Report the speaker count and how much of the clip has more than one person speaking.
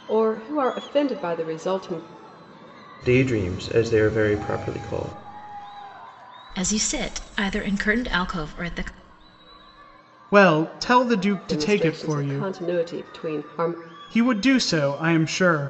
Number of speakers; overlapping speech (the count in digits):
4, about 7%